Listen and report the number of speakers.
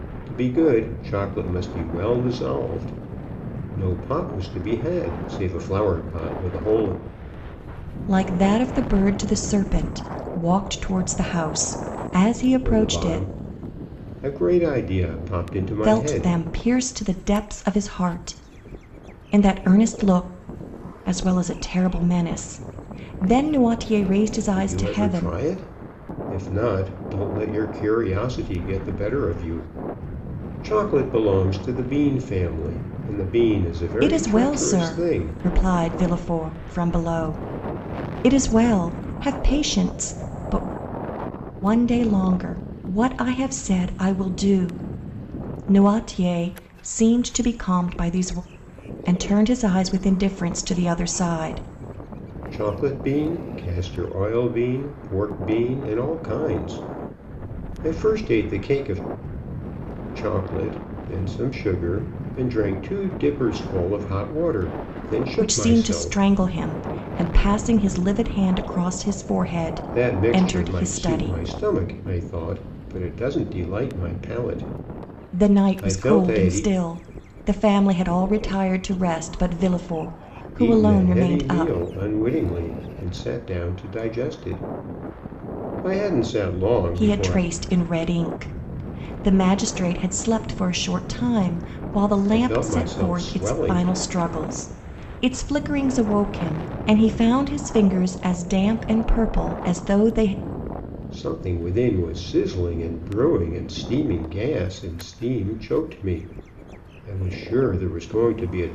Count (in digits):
2